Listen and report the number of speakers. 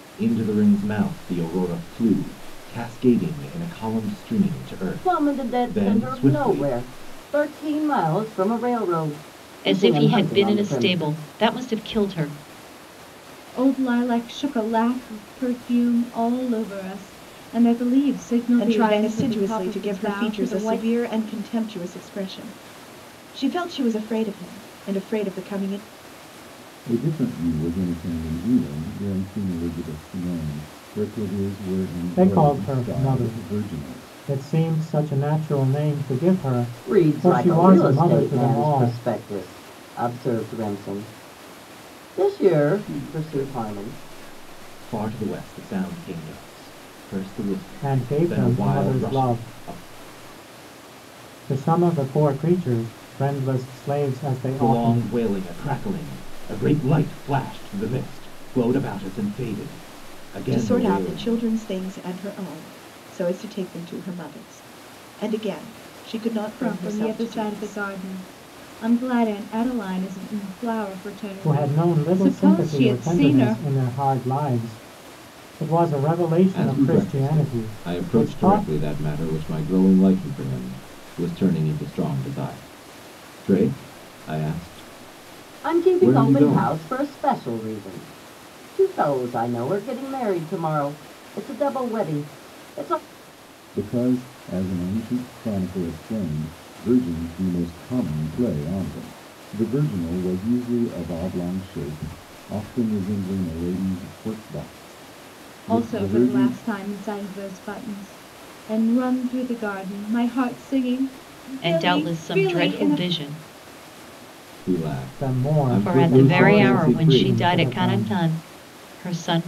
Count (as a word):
seven